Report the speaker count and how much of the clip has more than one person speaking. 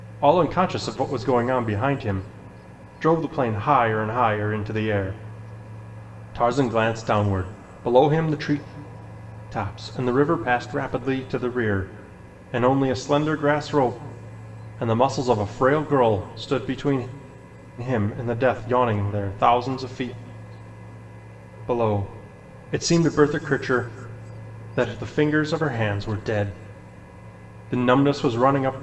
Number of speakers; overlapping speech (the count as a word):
one, no overlap